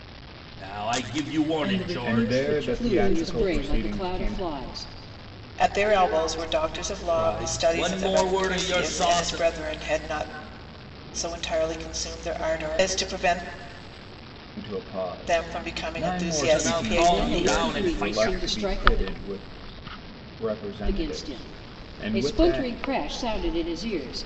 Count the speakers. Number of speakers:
five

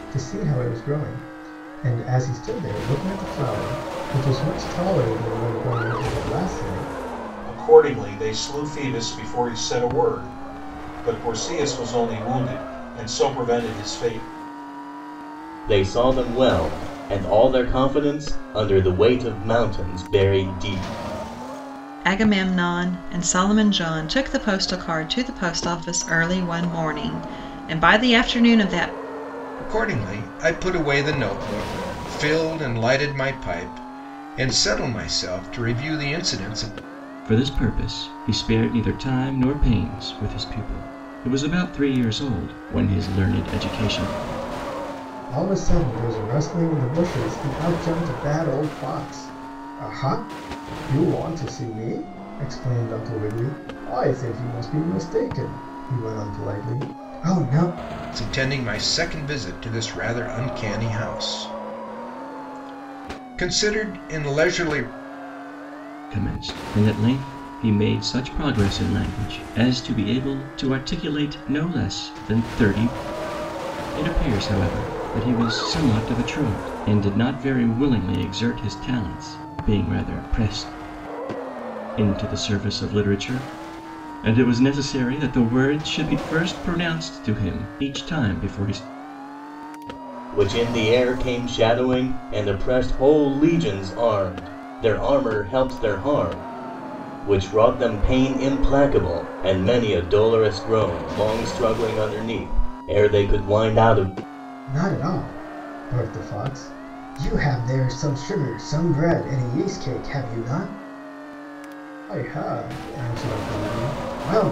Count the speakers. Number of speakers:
six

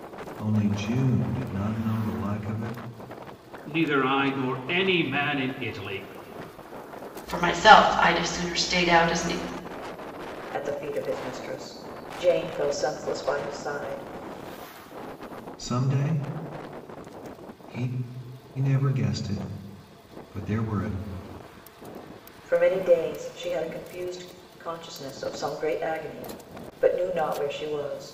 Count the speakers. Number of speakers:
four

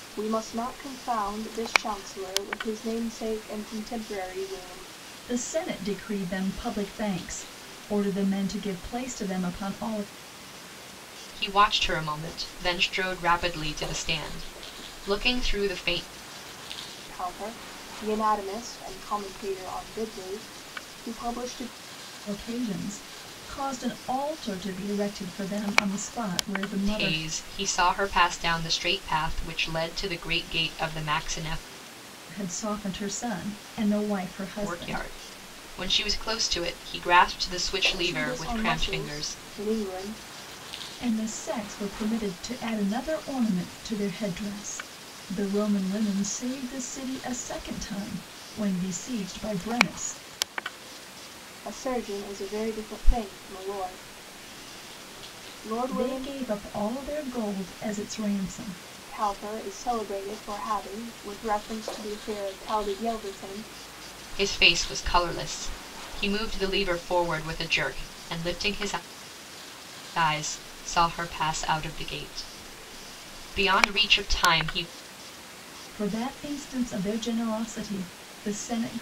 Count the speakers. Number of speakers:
three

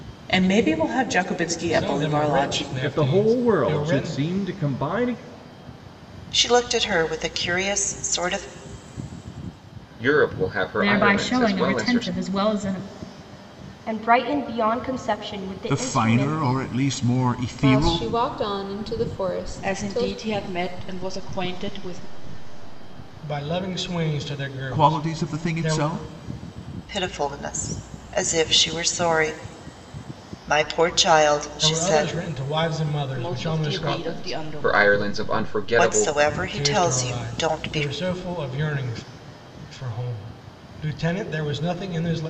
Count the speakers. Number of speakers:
ten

